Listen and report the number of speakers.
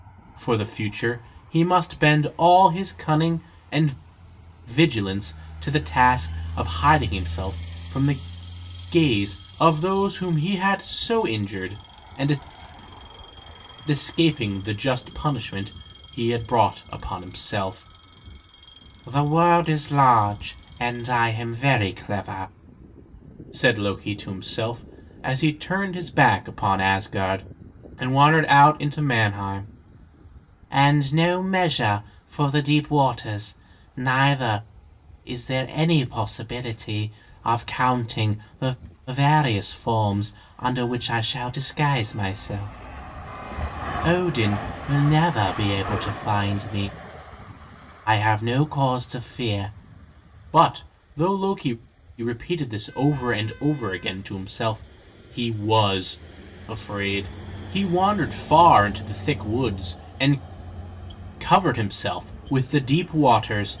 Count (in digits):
1